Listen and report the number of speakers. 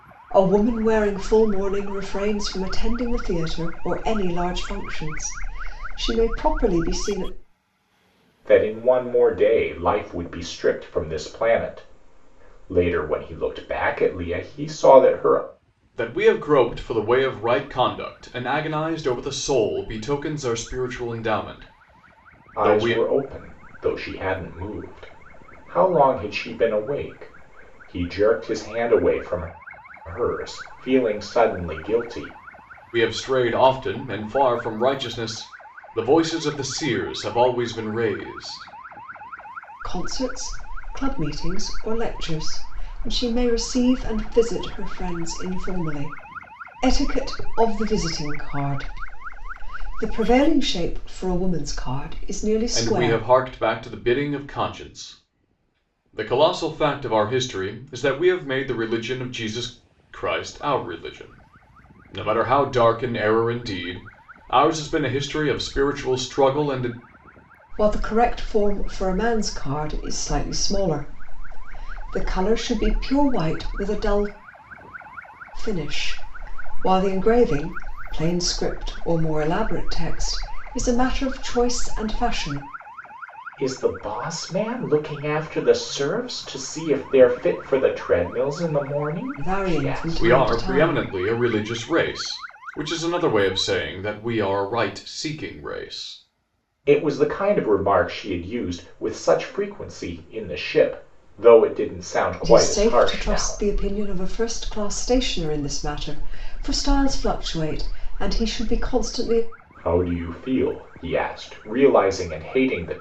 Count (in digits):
3